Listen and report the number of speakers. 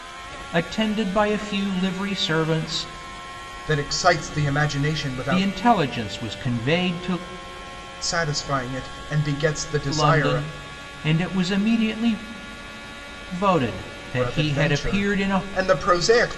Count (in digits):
2